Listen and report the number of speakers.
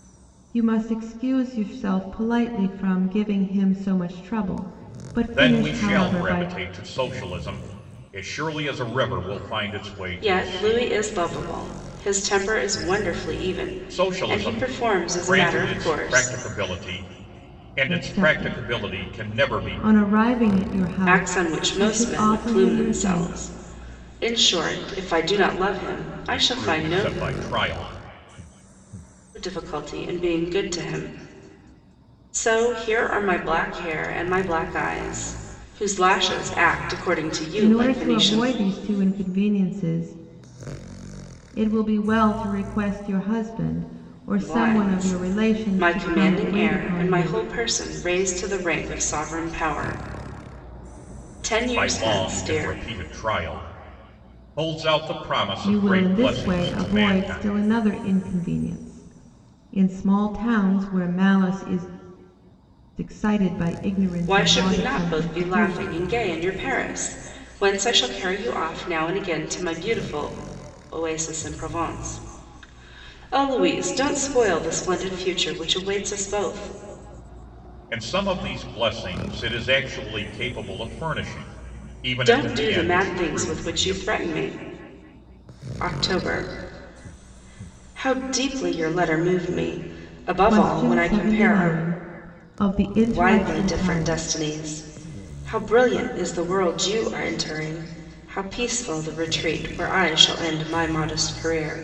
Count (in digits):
3